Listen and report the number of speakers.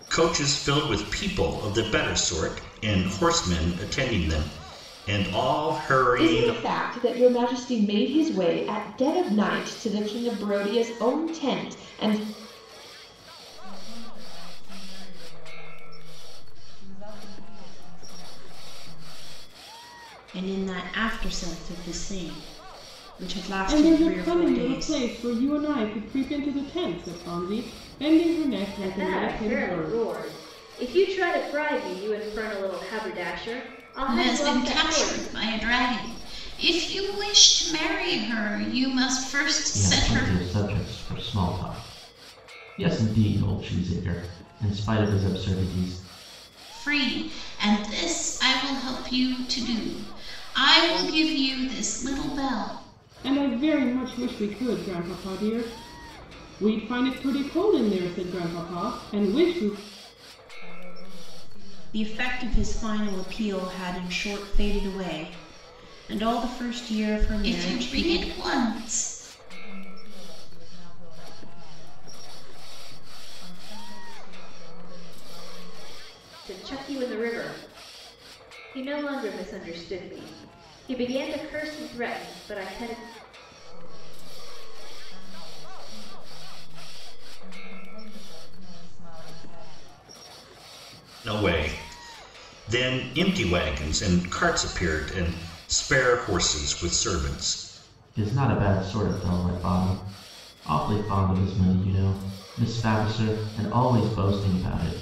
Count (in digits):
8